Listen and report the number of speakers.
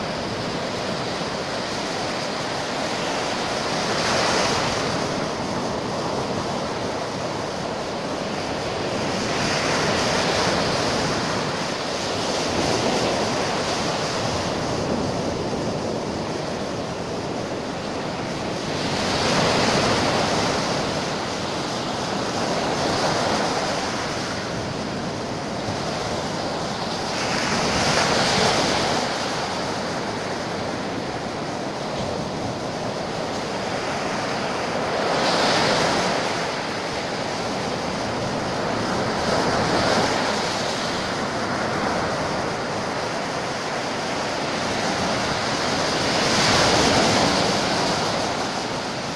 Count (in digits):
0